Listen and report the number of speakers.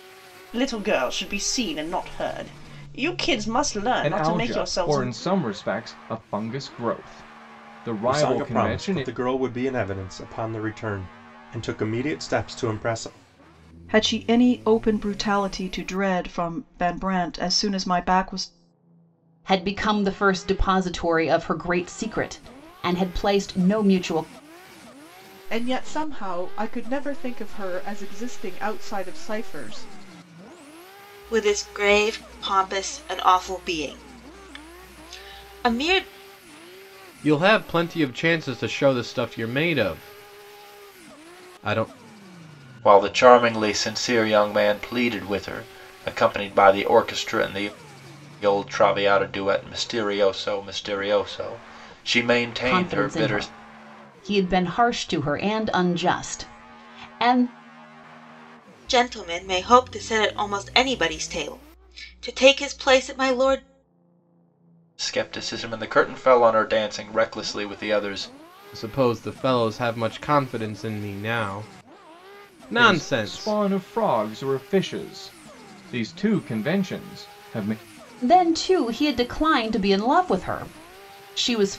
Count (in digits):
9